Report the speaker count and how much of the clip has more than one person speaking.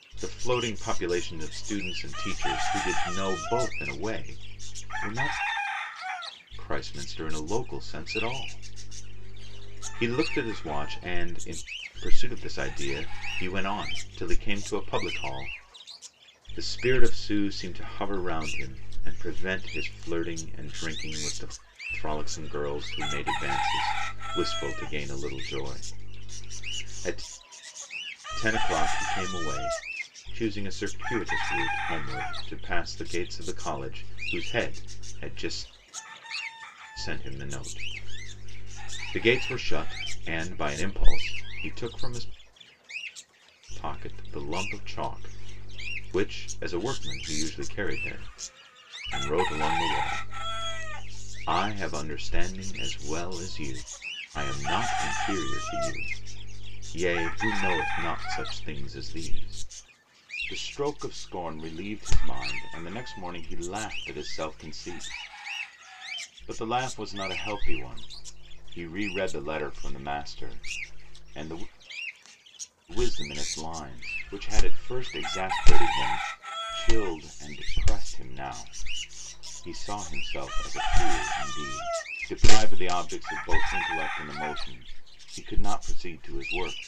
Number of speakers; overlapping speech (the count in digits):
1, no overlap